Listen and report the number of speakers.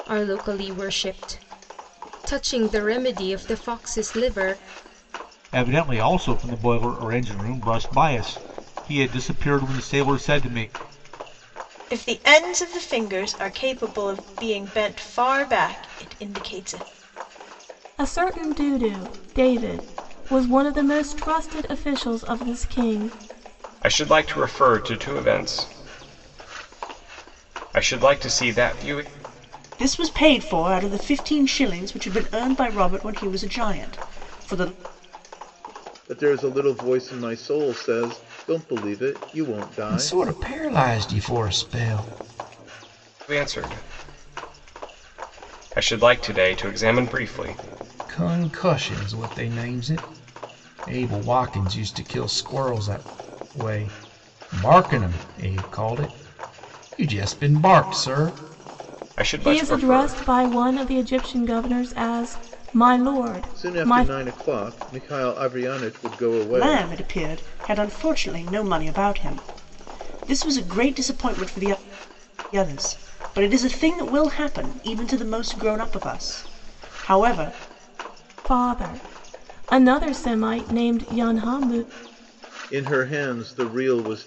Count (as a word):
eight